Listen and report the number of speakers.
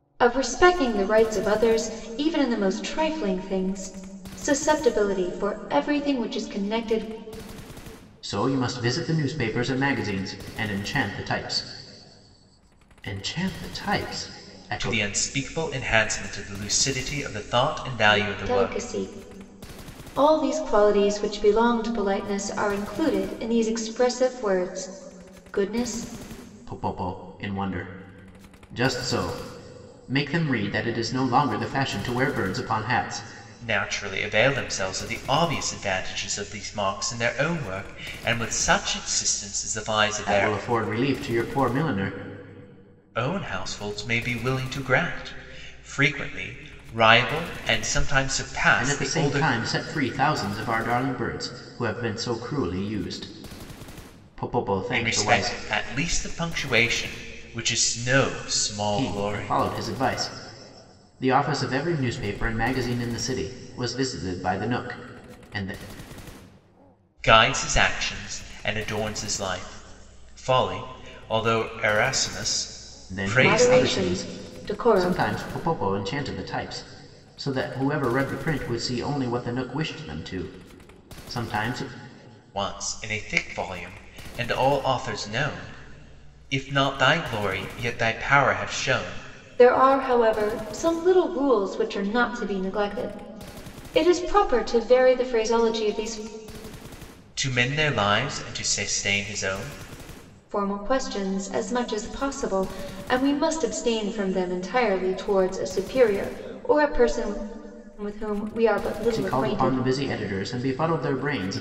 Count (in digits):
3